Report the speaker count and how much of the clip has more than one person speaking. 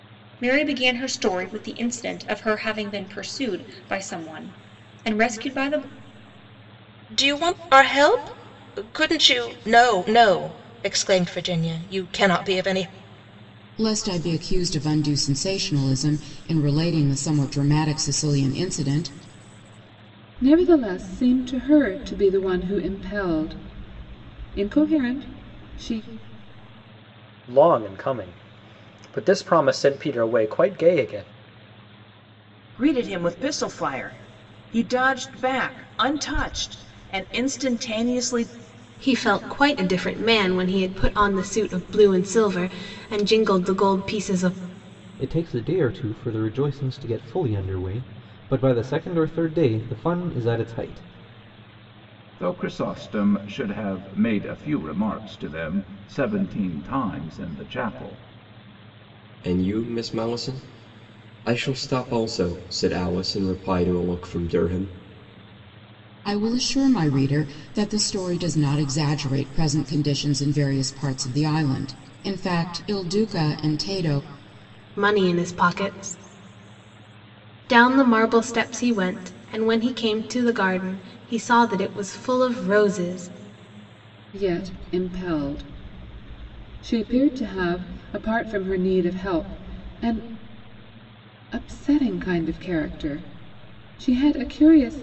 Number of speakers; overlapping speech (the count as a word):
ten, no overlap